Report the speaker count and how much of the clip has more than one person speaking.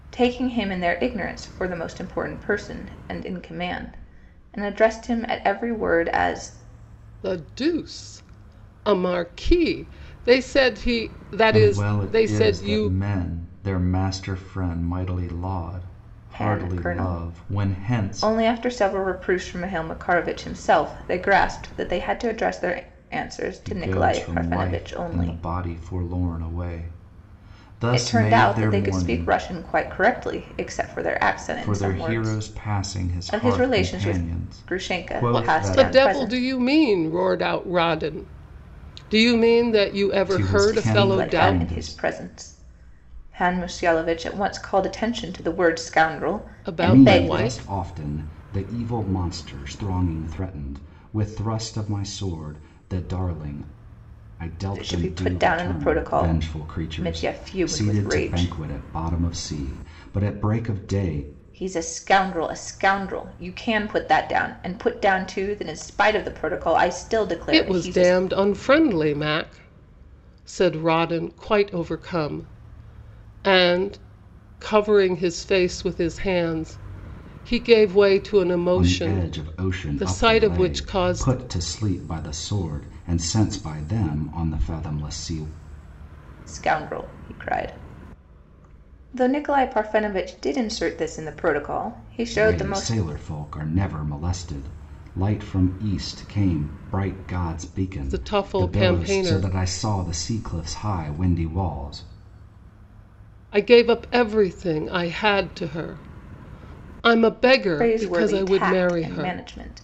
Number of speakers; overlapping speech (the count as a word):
three, about 23%